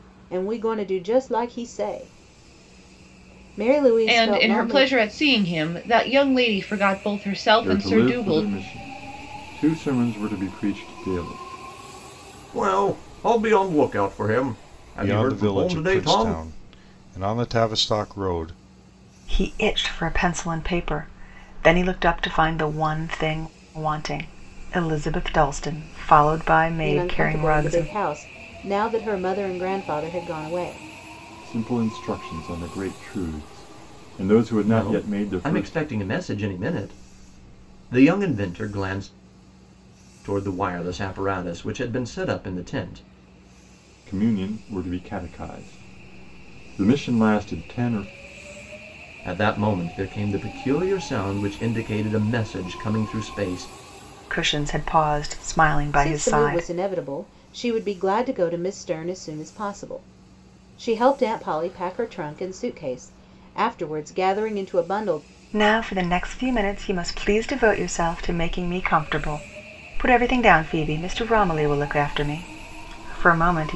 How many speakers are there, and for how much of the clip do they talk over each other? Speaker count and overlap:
six, about 9%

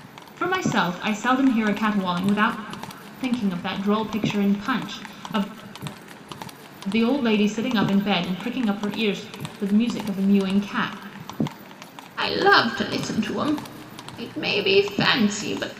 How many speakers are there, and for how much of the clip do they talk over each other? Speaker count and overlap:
one, no overlap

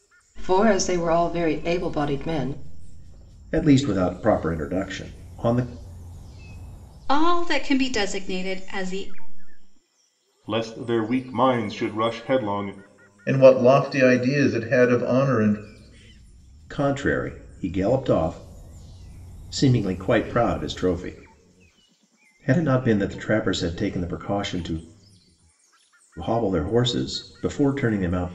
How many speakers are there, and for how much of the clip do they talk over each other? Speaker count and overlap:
five, no overlap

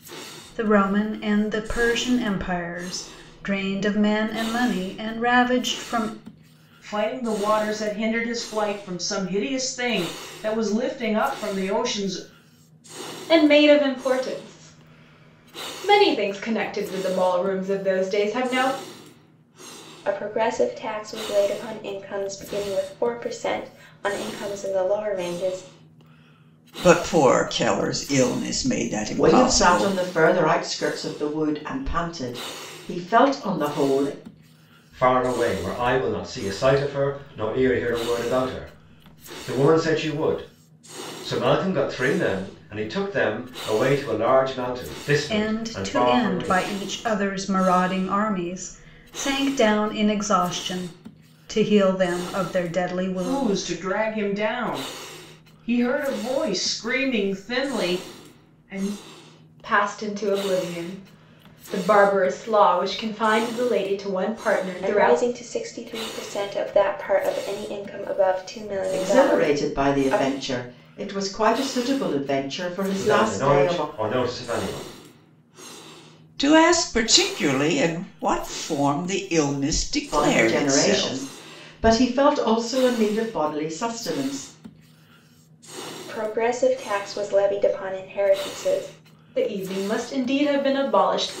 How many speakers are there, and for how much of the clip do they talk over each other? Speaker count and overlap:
seven, about 8%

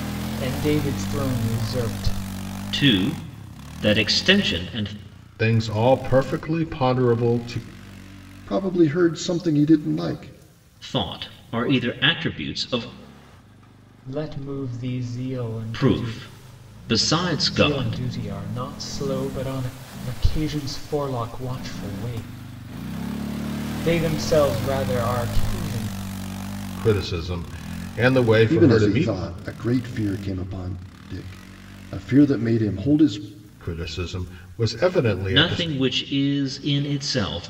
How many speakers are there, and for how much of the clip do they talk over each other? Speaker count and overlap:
four, about 6%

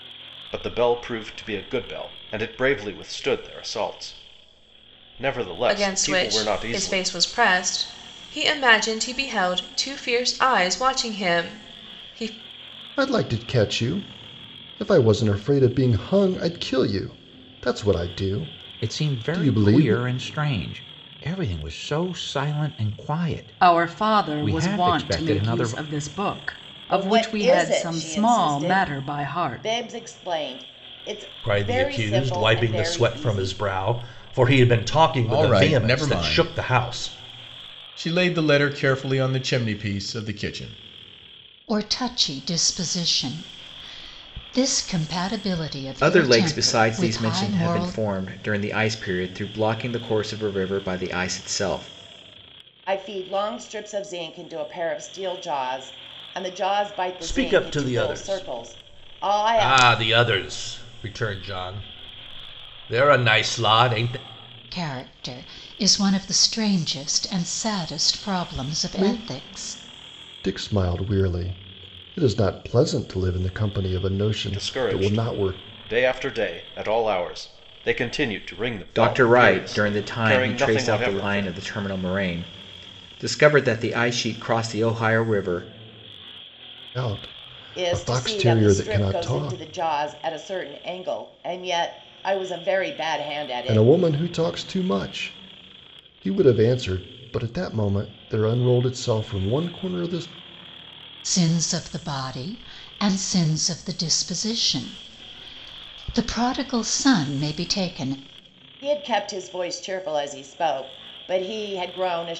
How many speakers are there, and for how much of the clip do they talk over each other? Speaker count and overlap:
ten, about 22%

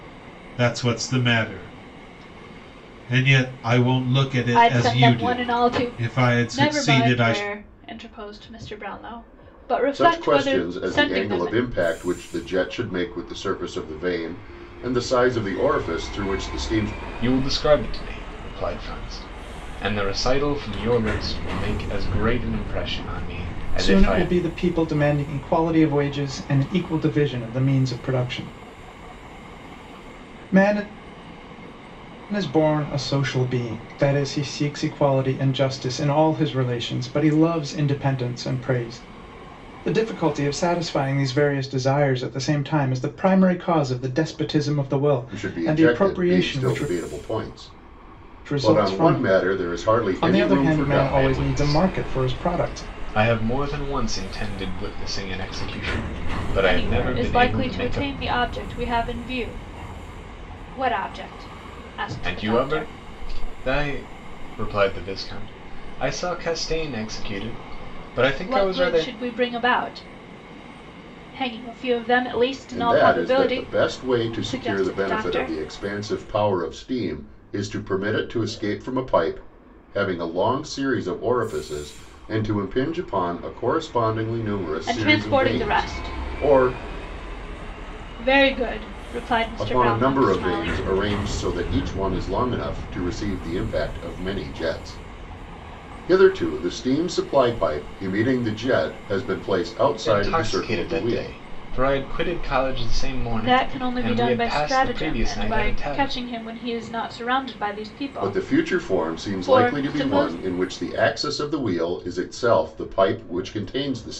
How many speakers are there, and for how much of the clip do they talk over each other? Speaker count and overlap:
five, about 23%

